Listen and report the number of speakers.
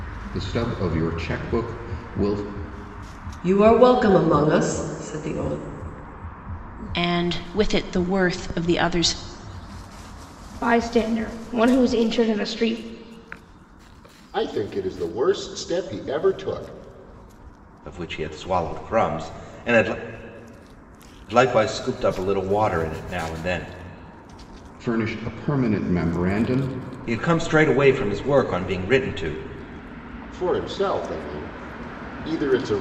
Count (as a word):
six